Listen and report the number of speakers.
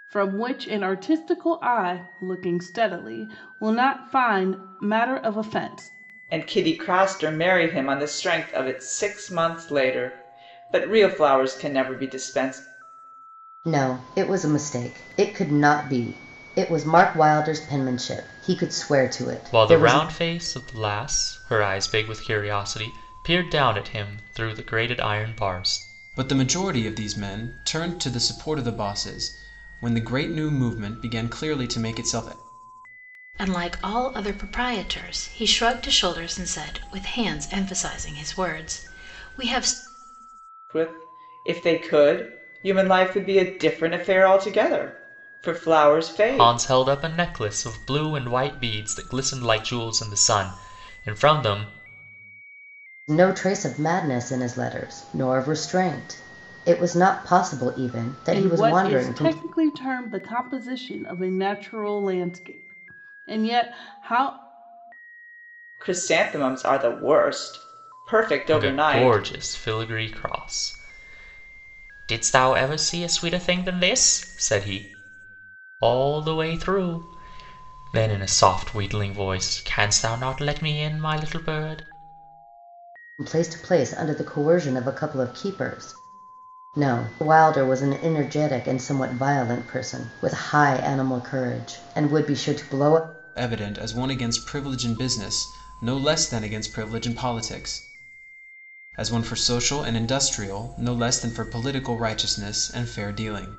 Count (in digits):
6